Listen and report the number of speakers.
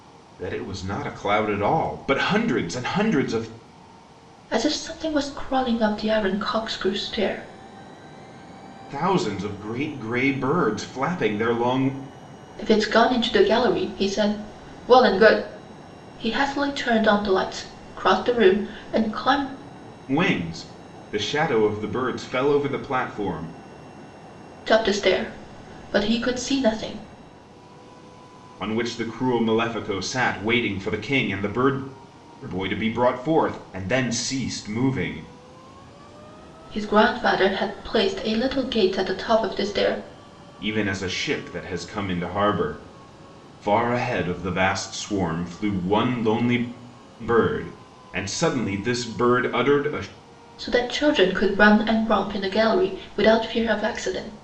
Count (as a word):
two